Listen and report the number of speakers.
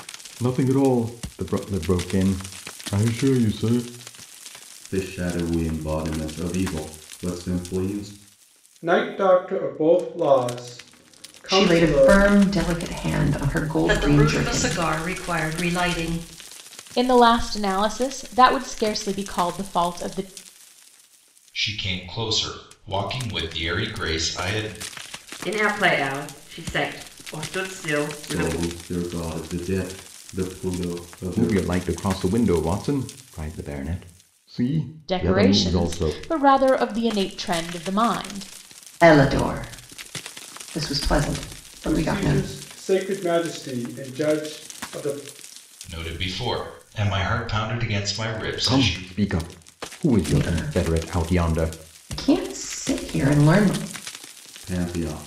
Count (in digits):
8